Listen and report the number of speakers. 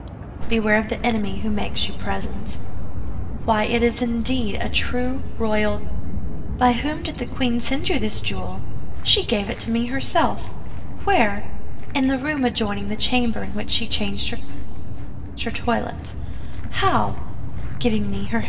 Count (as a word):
one